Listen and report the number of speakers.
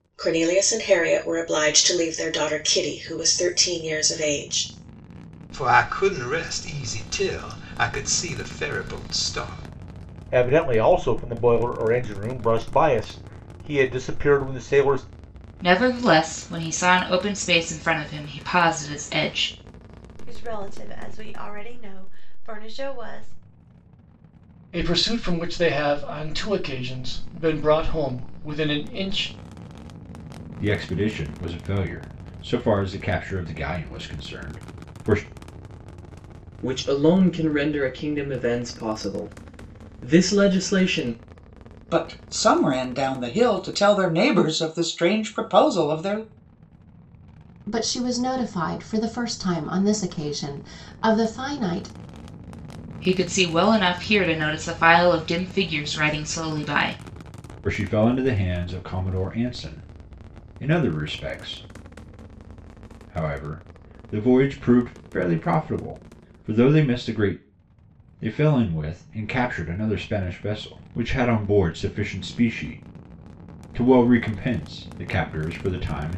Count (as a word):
ten